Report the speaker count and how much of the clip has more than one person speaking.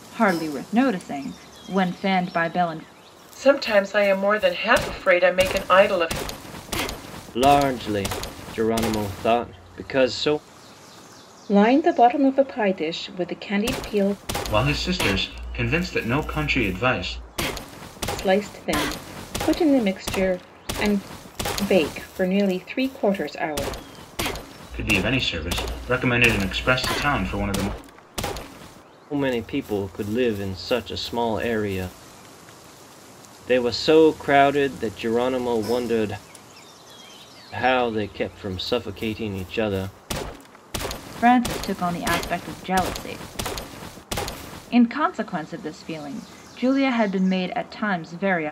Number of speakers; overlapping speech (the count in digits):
5, no overlap